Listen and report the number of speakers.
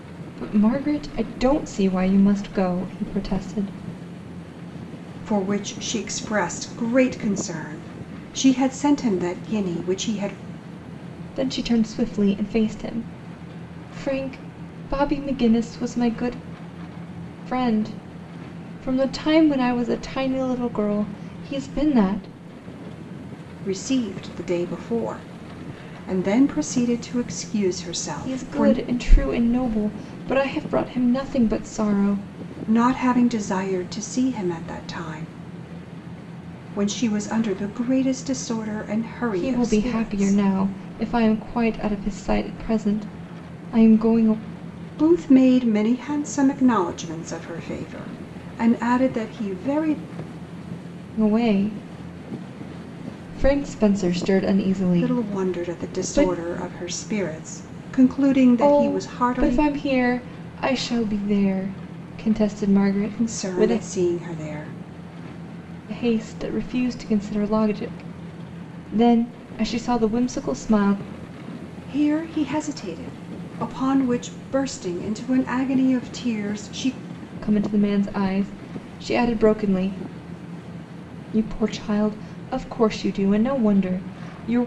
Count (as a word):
two